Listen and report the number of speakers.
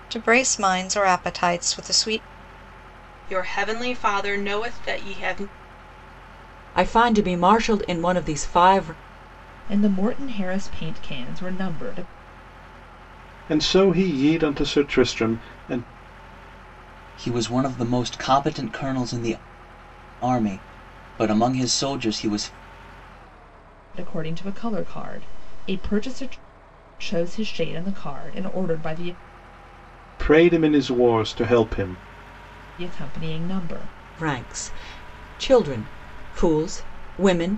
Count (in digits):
6